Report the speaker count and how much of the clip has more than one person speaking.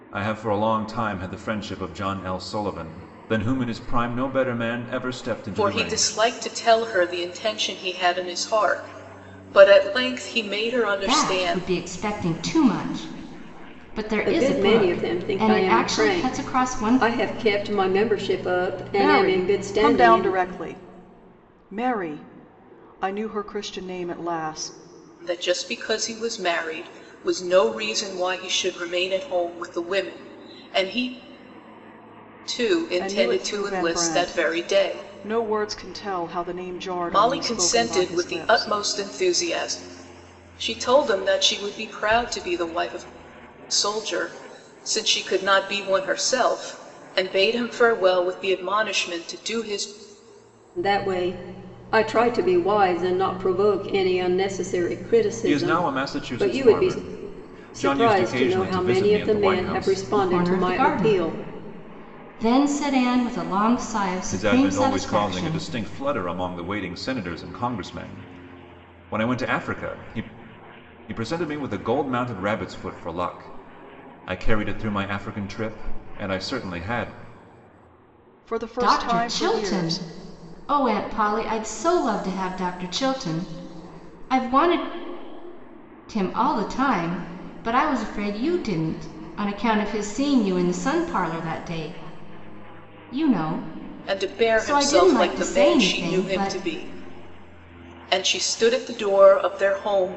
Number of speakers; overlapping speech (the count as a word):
five, about 20%